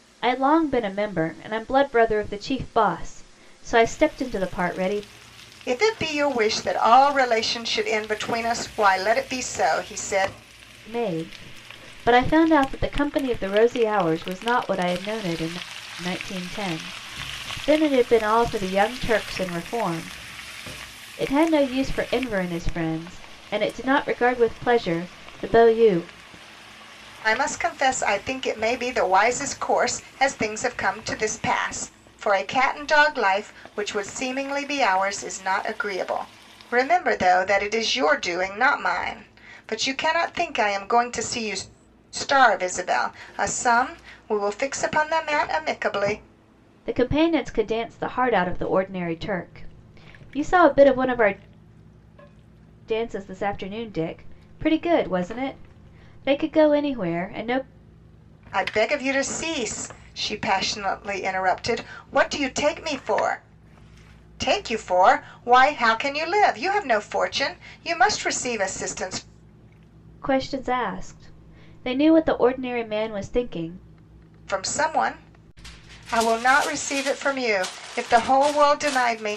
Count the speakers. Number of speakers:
2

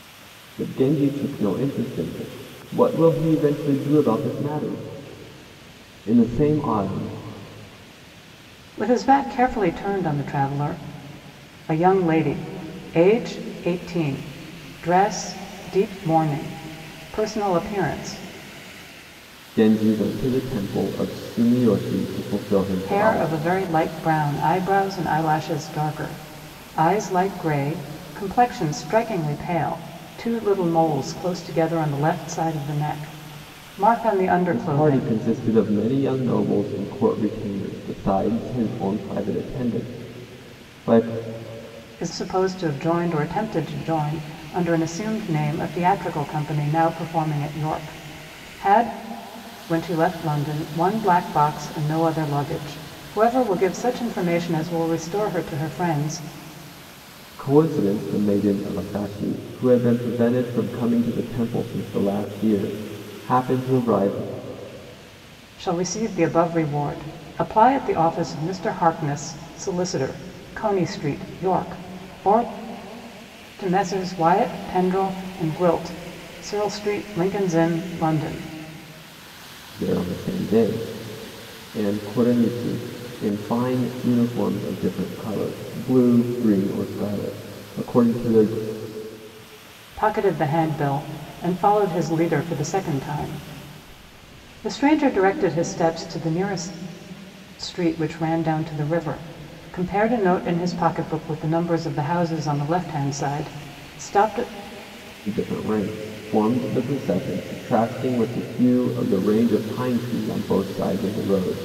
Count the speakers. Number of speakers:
2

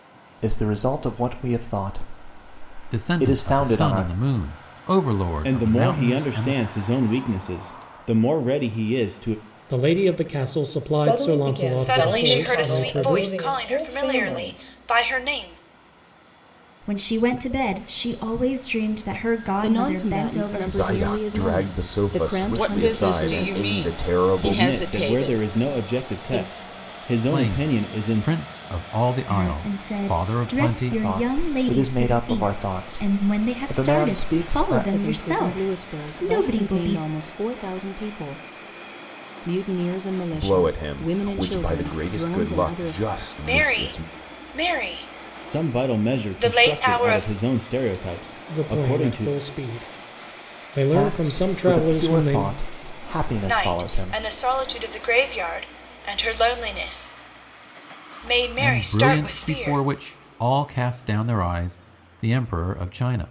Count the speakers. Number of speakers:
10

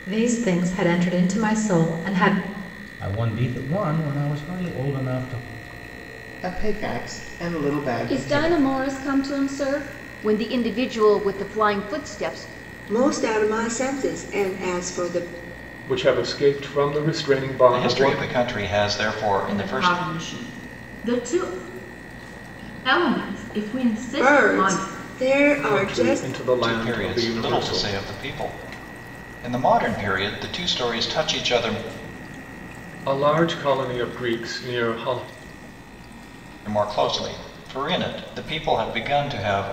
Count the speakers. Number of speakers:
9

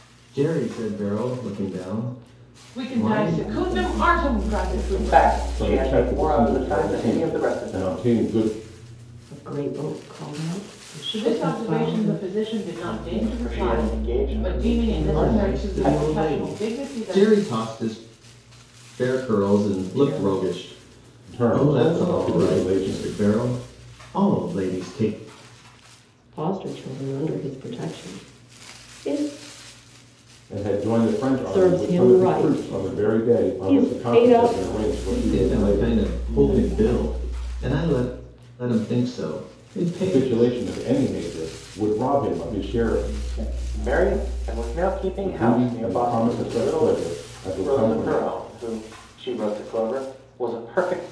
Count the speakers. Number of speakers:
6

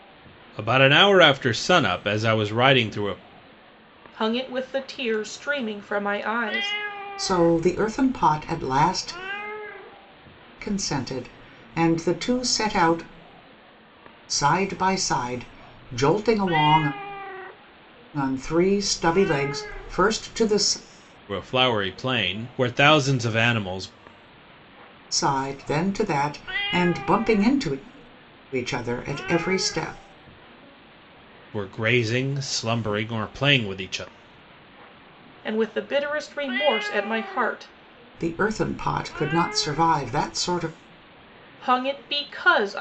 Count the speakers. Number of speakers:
3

